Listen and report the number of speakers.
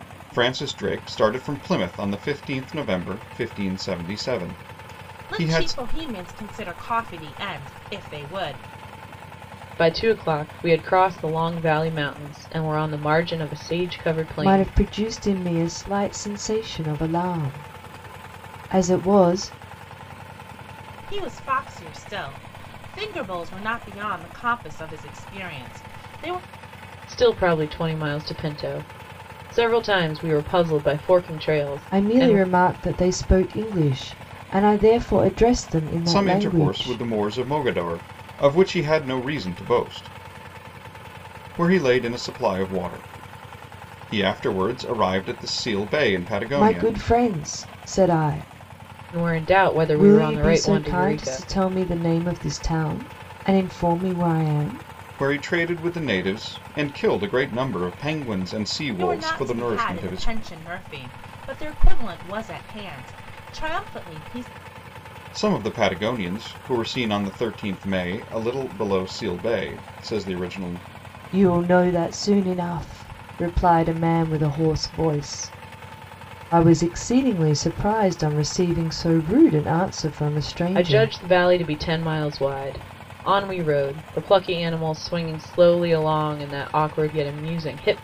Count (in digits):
4